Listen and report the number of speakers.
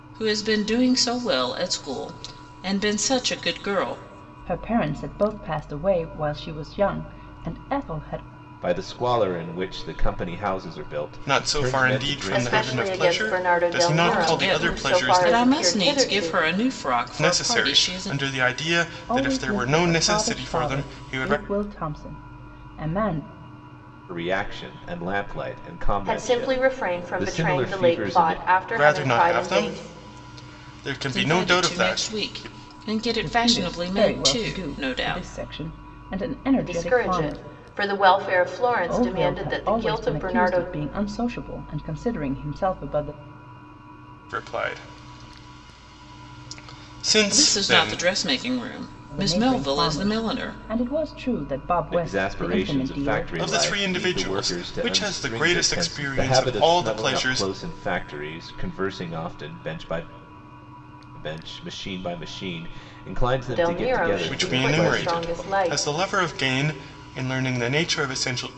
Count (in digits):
5